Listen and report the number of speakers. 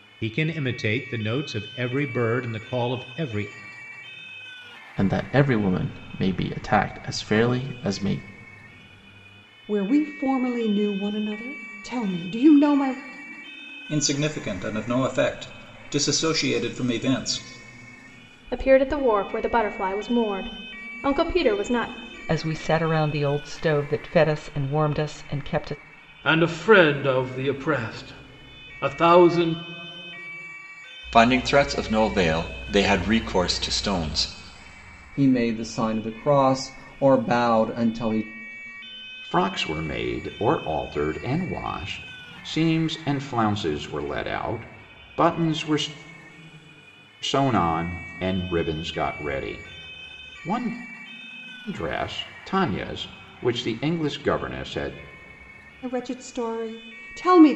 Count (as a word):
ten